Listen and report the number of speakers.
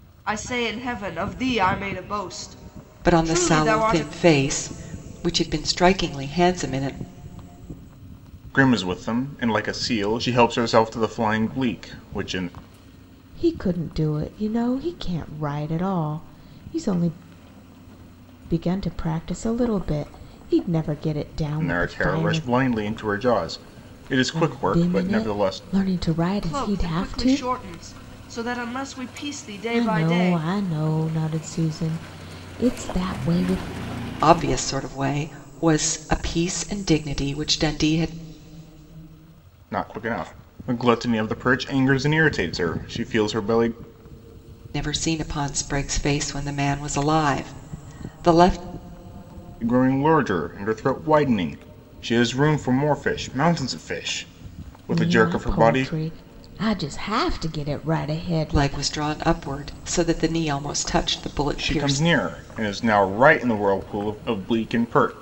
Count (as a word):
four